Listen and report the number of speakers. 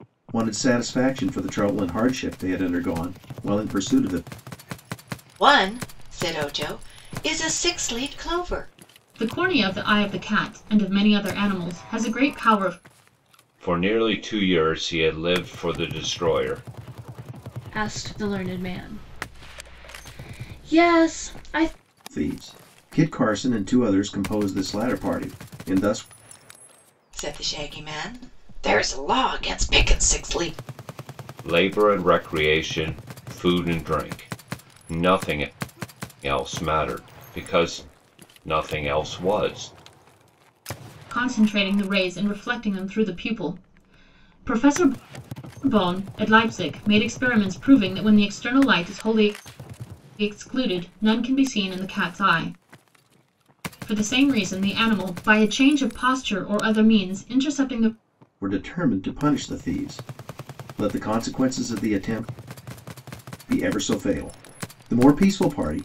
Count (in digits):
5